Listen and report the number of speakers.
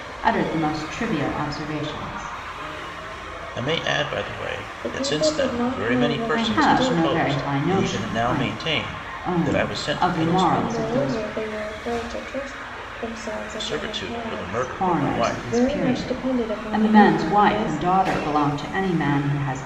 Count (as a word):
three